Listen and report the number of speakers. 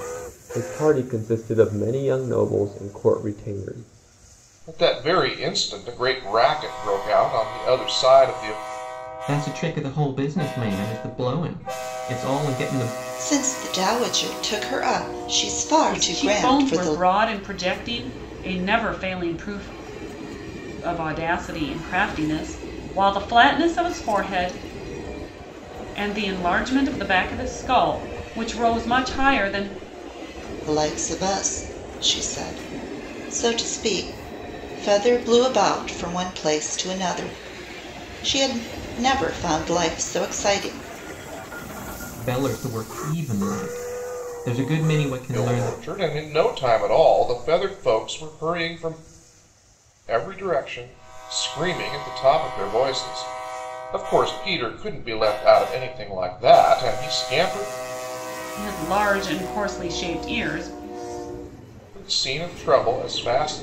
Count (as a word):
five